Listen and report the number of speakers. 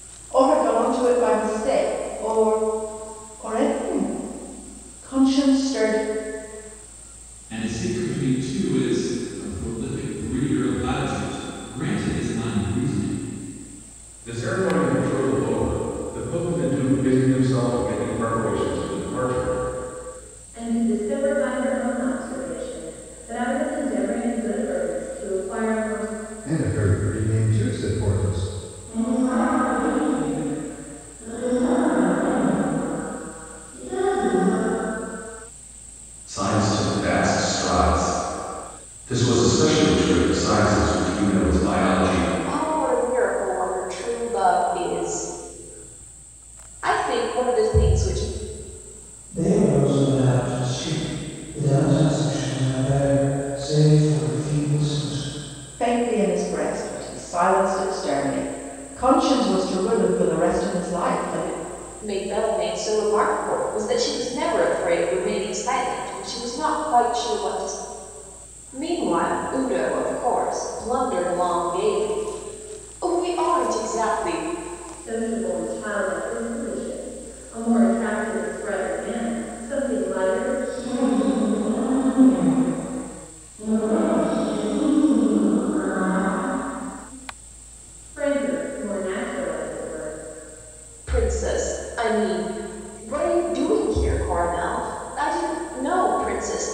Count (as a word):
nine